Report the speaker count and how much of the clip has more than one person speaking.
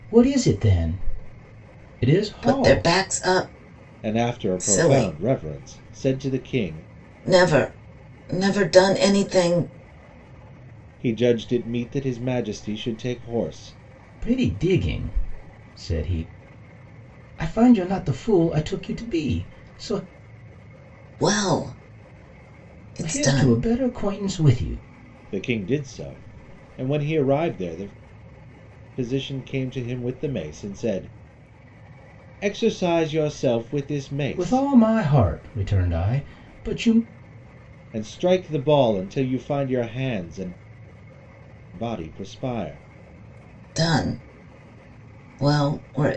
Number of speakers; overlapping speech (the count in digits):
3, about 6%